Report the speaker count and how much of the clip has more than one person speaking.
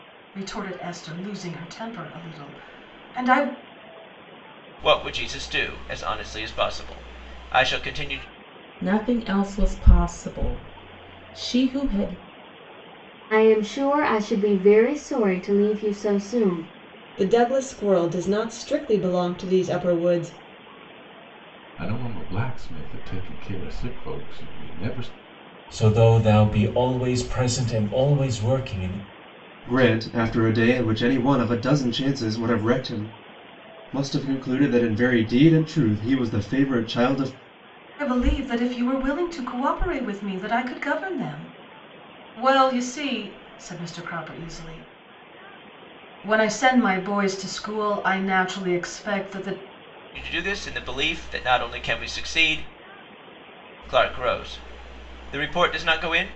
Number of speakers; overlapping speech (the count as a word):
eight, no overlap